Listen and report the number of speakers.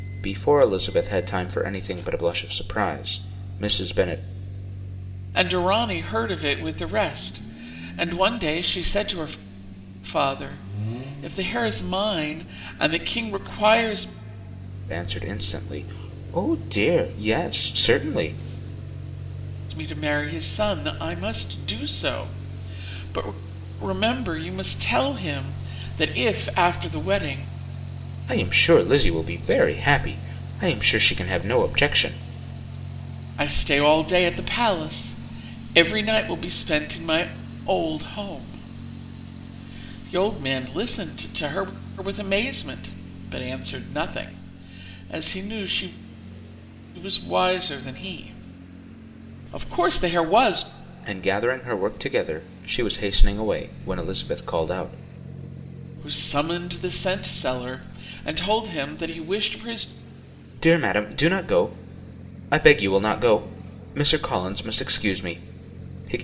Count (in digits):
2